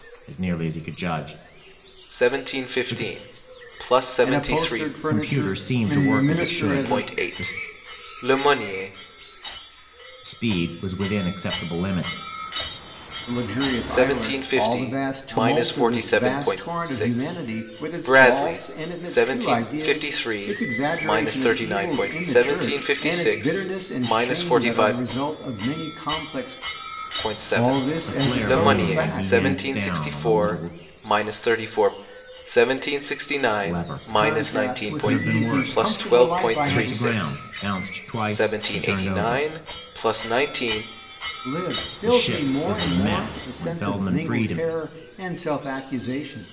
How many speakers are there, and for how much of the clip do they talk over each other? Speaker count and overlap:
3, about 56%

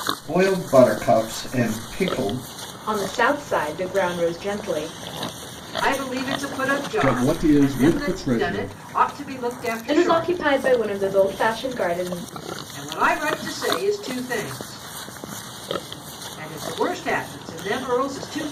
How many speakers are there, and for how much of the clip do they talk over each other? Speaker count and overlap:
4, about 13%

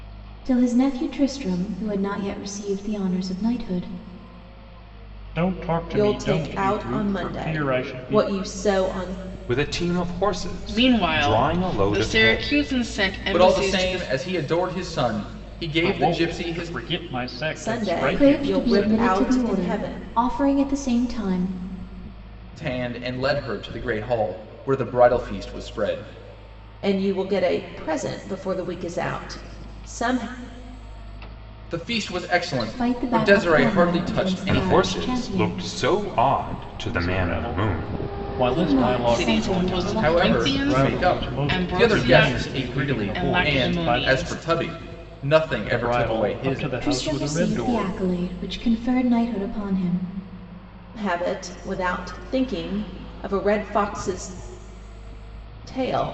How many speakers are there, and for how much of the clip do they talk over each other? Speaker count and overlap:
6, about 38%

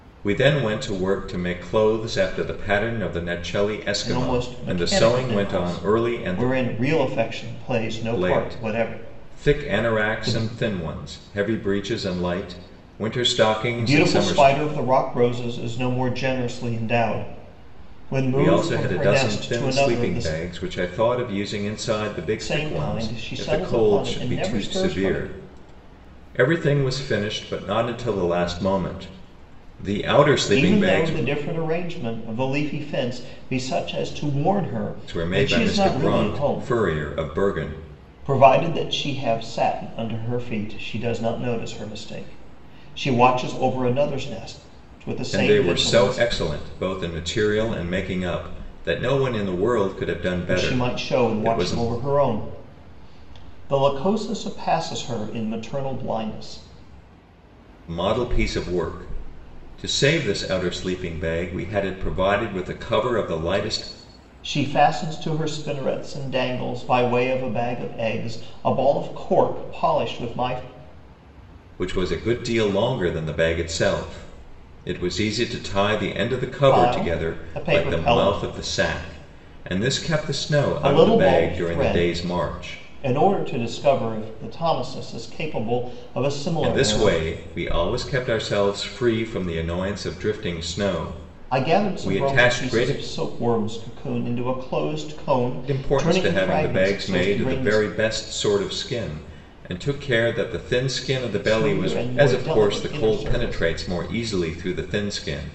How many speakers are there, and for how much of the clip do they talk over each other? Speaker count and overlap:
2, about 24%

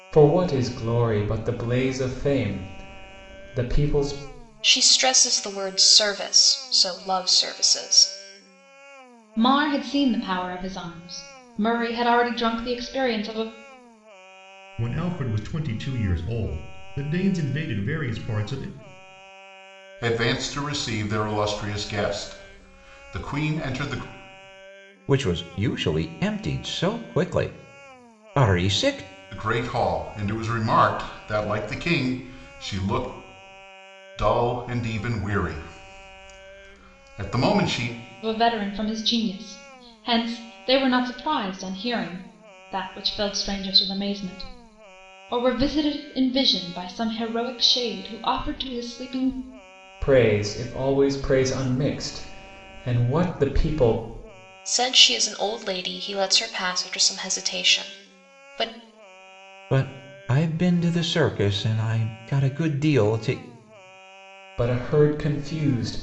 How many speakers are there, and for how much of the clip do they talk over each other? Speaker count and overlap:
6, no overlap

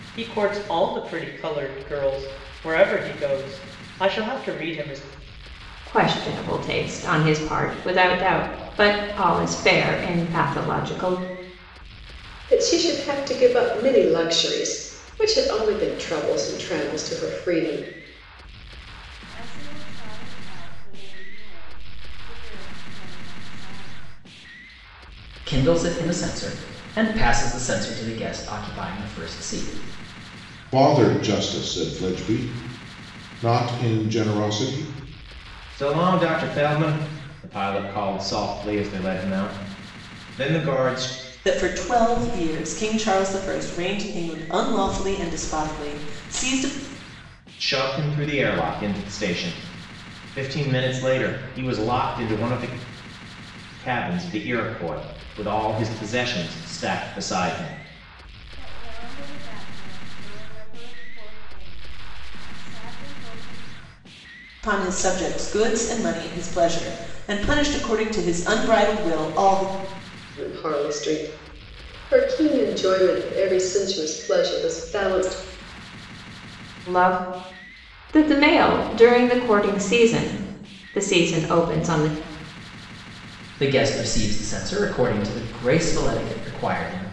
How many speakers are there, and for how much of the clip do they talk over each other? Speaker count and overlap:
8, no overlap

